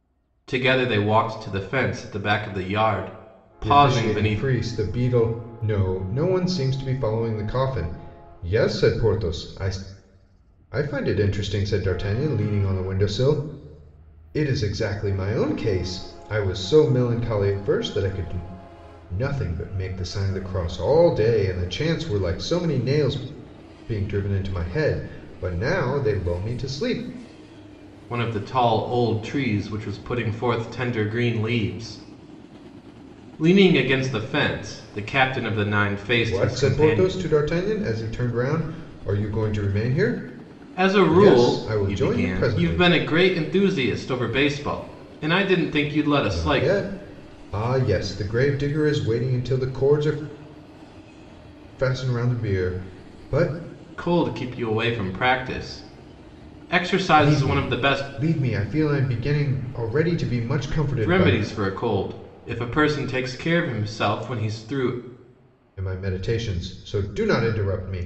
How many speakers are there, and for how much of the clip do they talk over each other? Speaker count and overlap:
two, about 8%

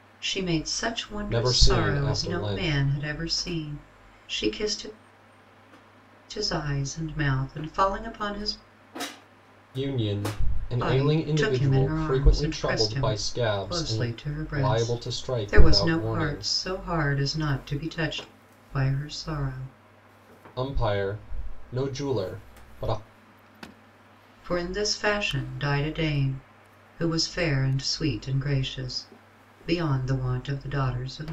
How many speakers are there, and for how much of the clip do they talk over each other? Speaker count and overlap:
two, about 20%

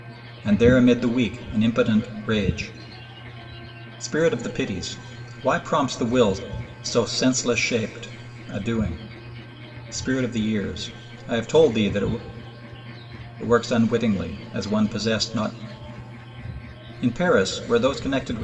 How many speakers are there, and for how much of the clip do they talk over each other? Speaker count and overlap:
one, no overlap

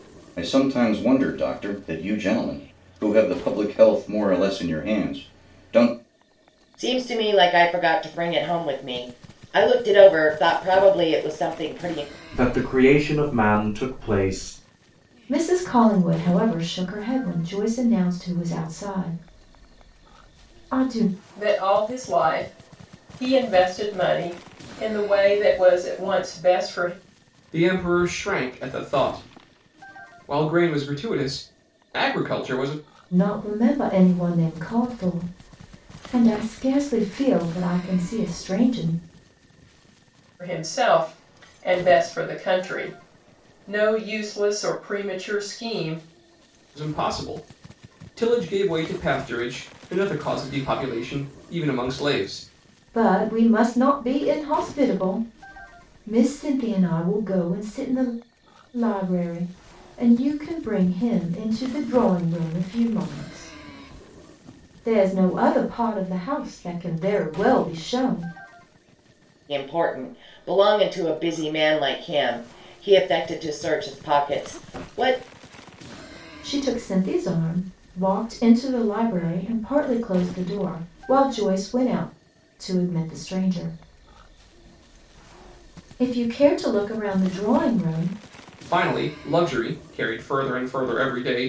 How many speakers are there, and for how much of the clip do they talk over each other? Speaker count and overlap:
six, no overlap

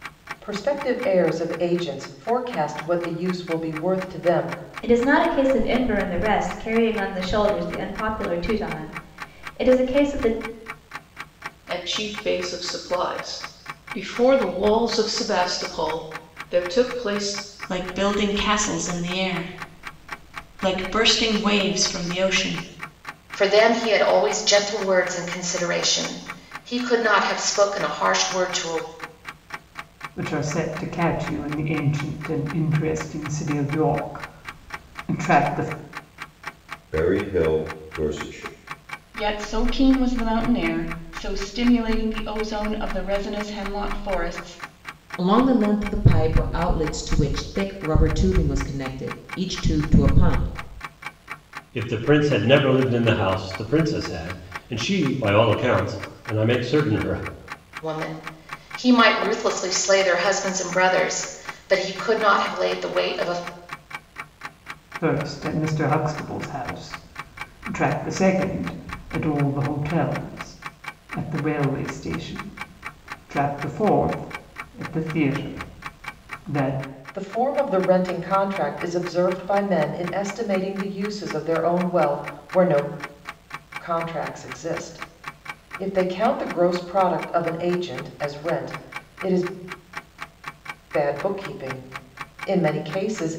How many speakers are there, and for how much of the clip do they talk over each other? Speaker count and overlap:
ten, no overlap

